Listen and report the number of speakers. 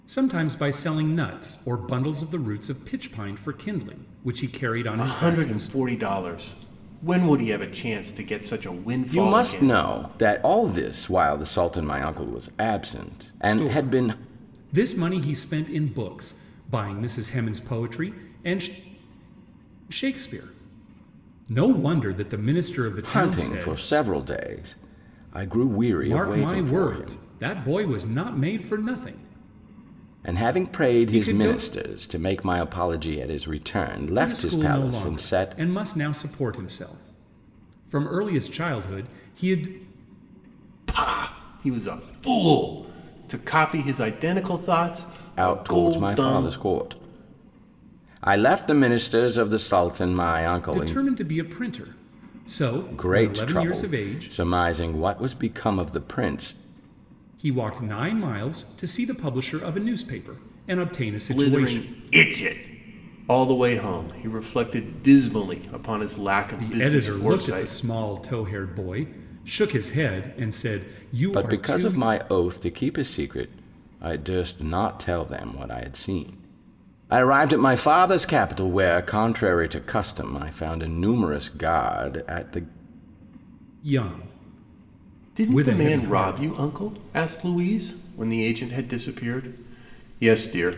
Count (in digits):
3